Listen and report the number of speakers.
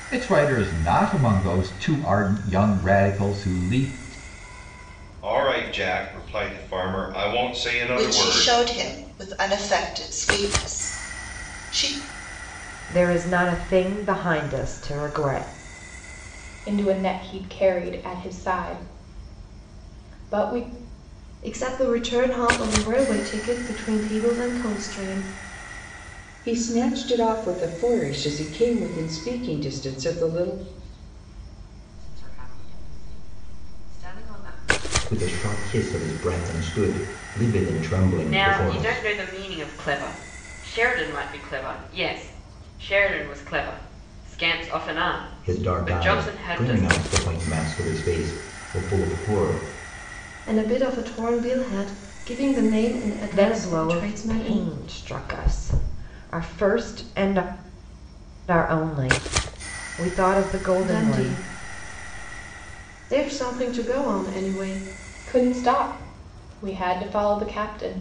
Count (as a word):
ten